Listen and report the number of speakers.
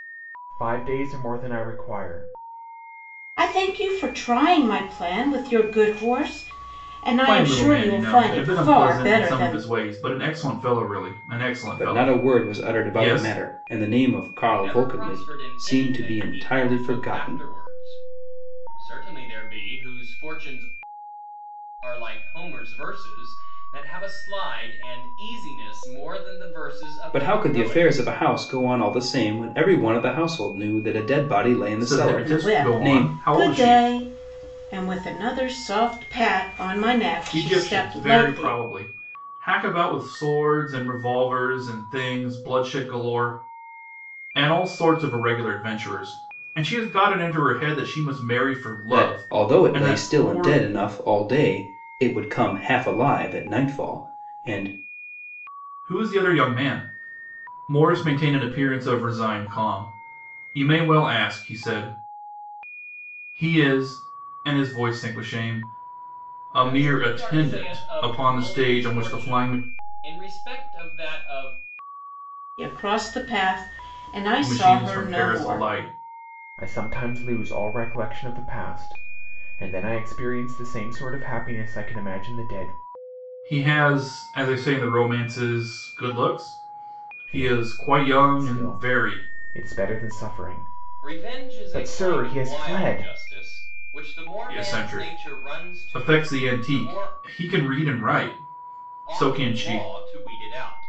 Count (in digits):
5